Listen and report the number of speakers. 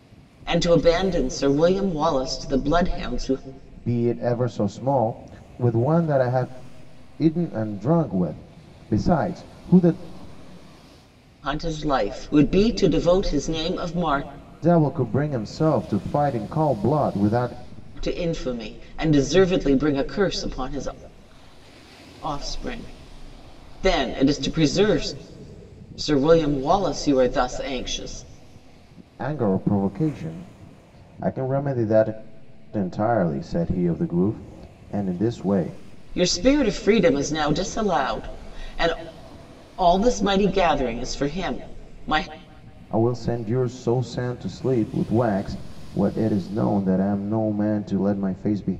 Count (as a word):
two